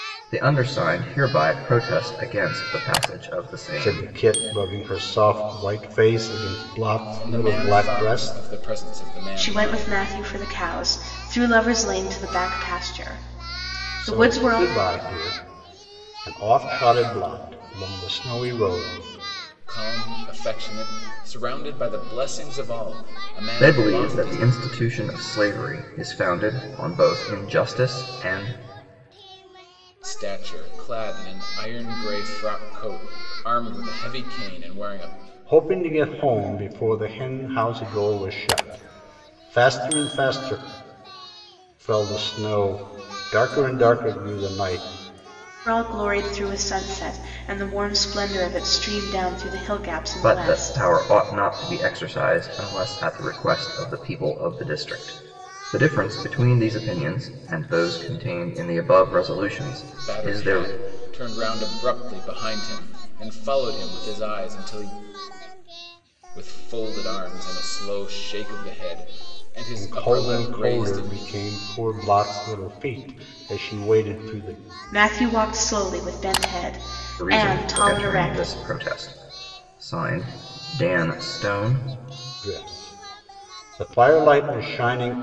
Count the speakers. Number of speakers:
4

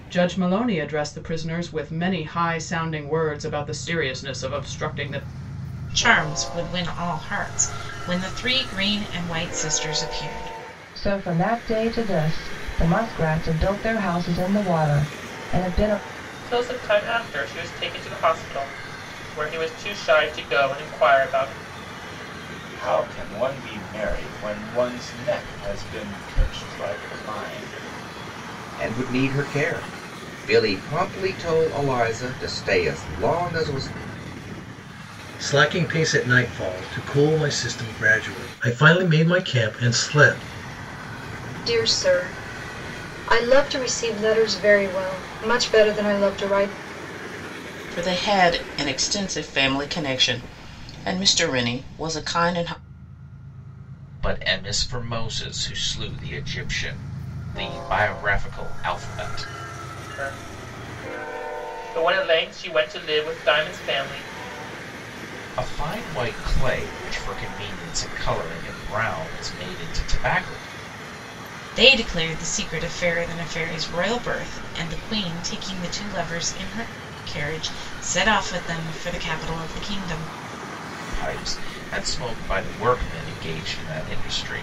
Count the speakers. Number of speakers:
10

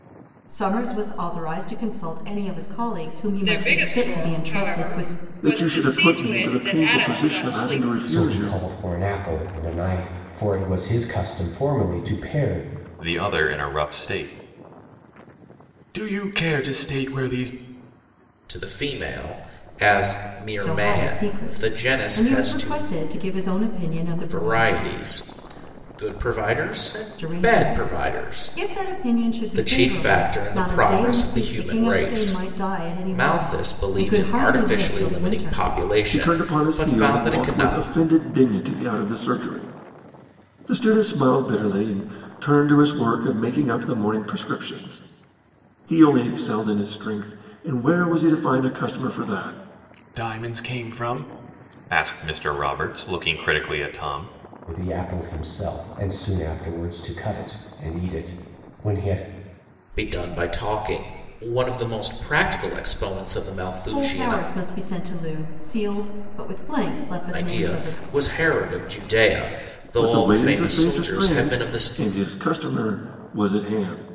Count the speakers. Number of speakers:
6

